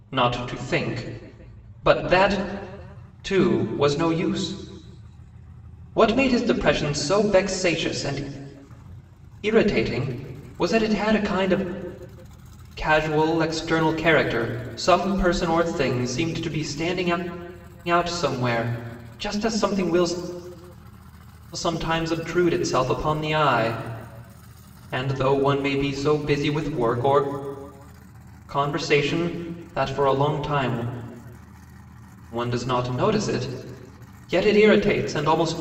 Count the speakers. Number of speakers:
one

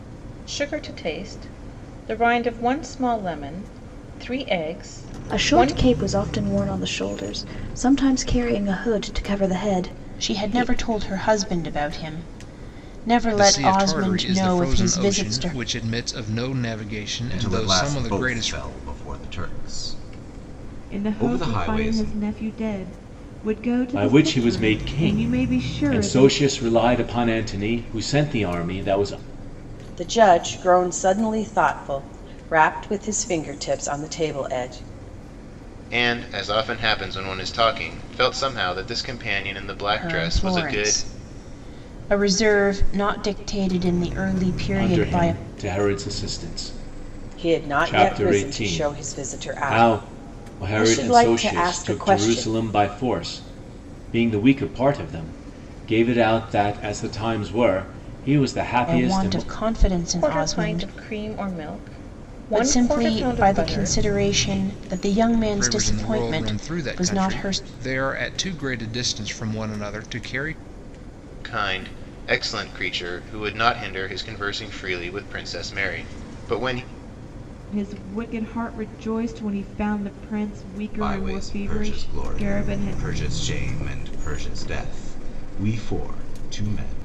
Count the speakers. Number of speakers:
nine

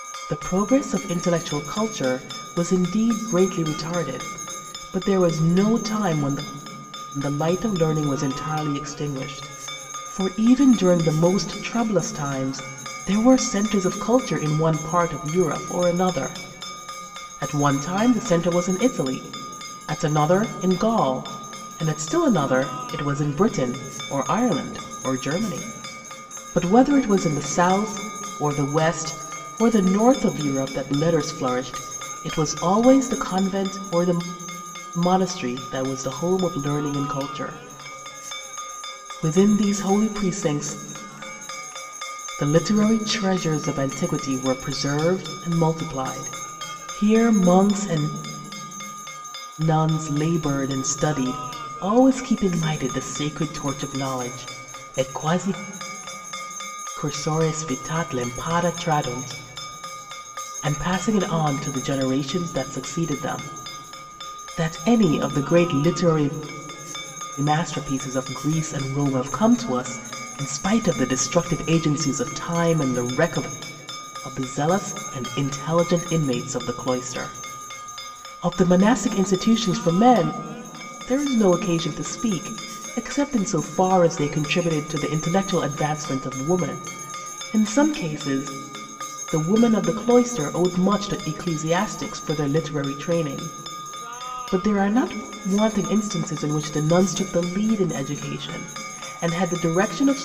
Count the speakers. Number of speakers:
one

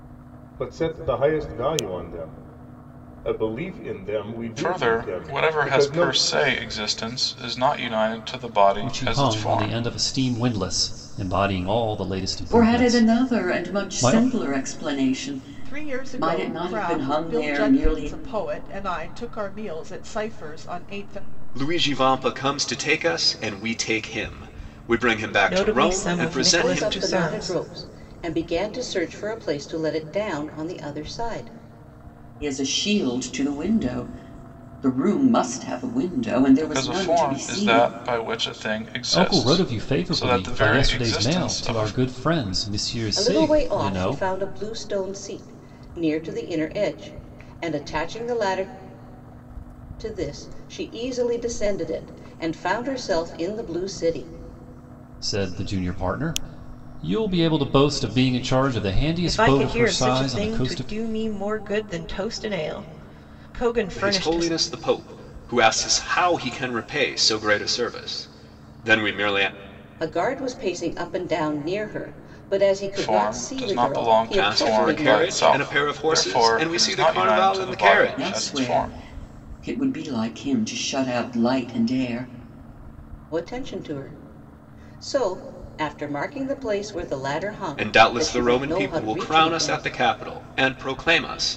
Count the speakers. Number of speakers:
eight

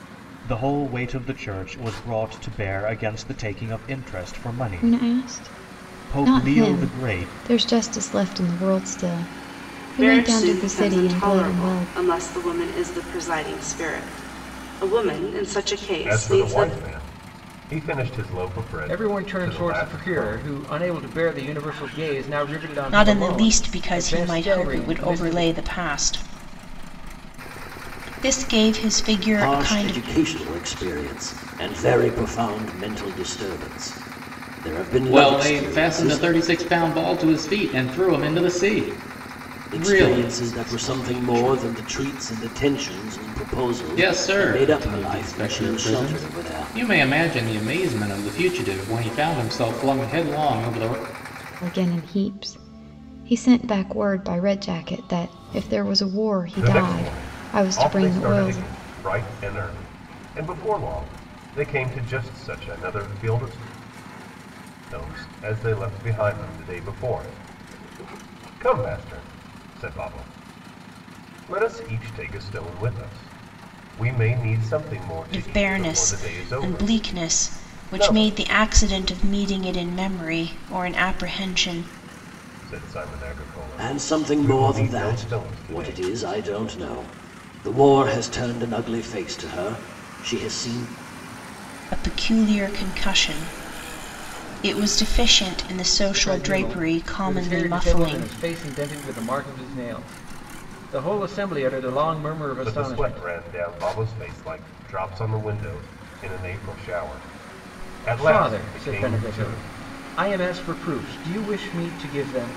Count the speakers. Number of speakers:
eight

